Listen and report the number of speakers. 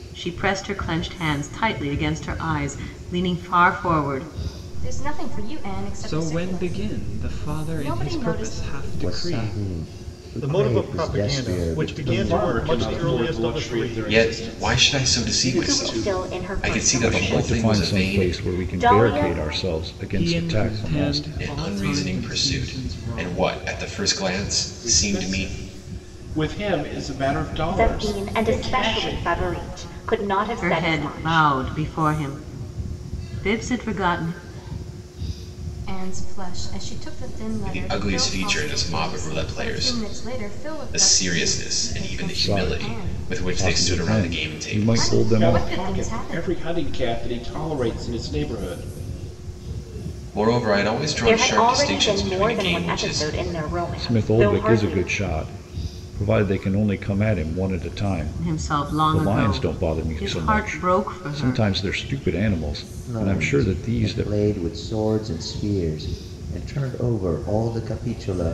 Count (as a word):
nine